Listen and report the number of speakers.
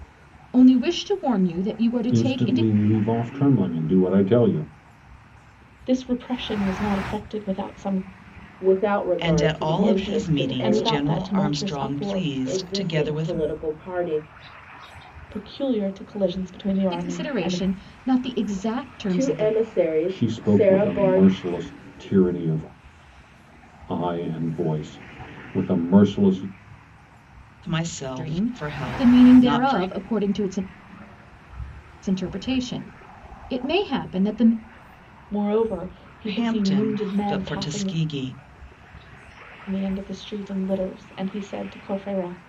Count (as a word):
five